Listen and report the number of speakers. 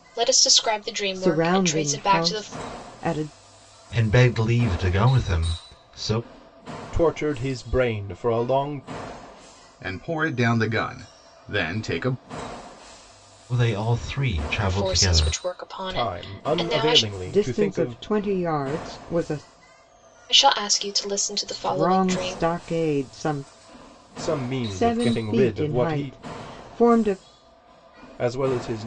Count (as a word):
five